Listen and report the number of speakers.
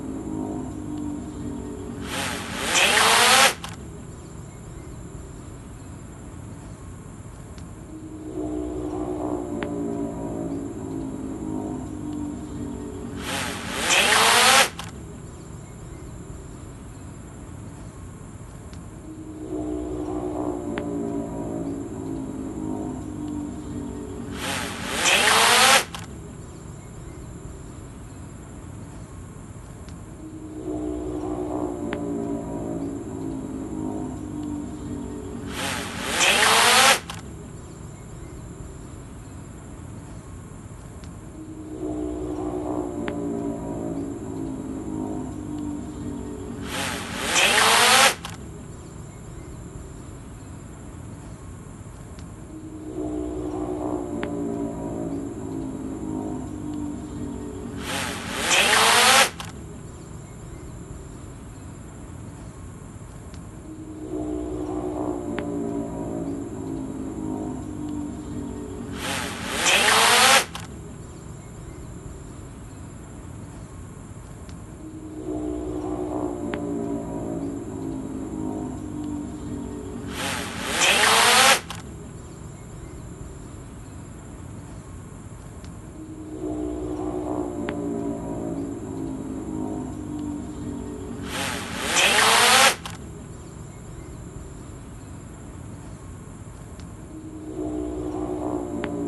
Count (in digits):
0